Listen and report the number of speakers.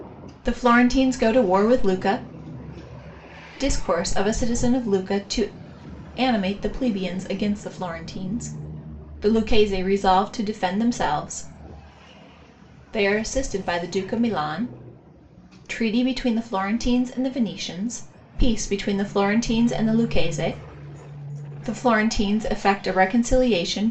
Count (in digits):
1